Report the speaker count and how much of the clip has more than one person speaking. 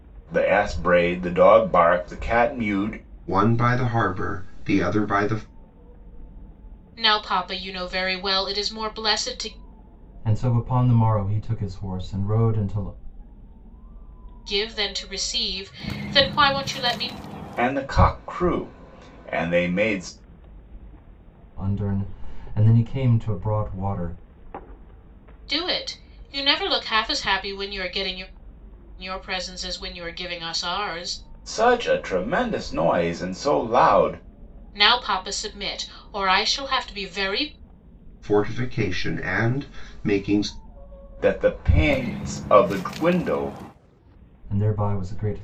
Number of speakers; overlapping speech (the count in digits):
4, no overlap